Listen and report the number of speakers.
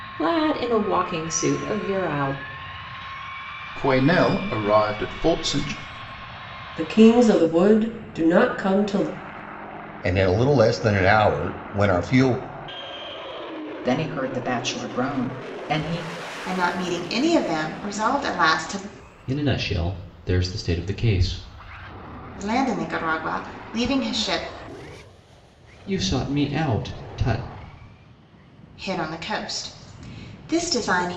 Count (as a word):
seven